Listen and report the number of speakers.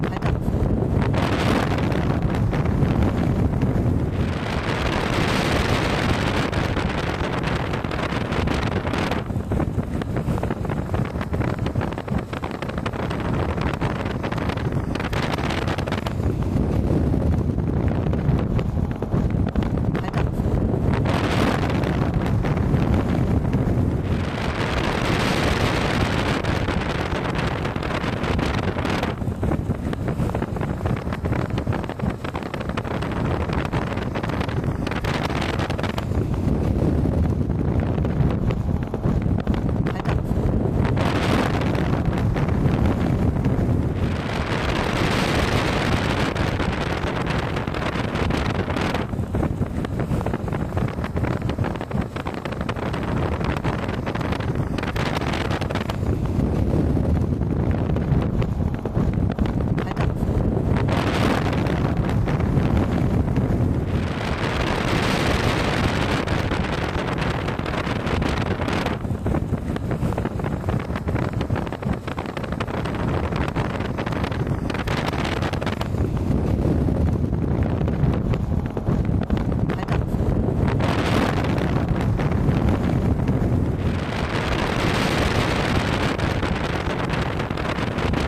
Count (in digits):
0